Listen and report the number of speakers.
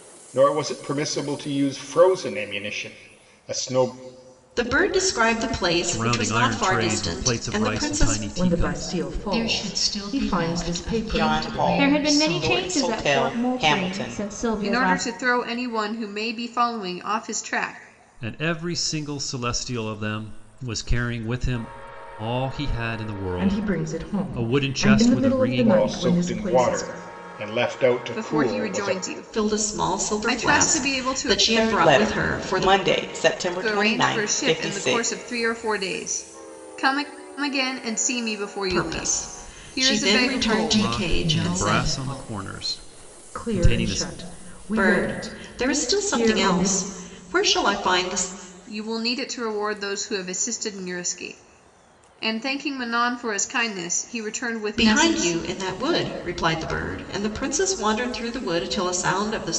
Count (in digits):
8